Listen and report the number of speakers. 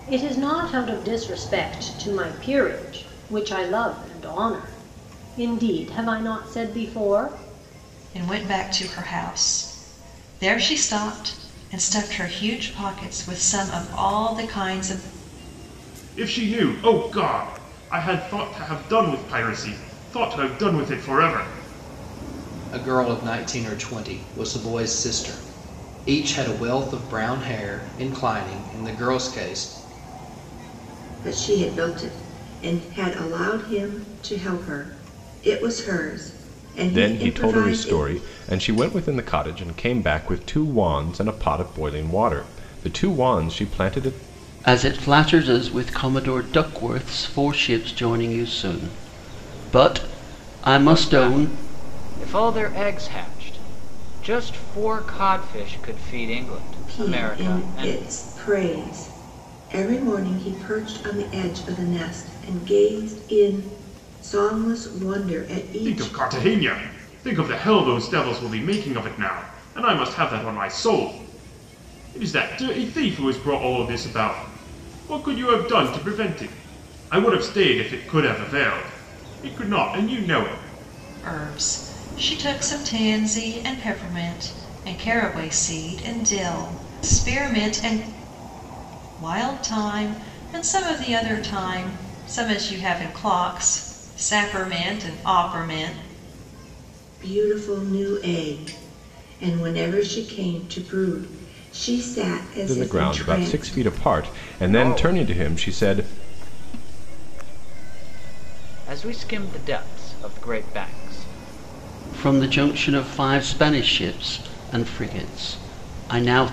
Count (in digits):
8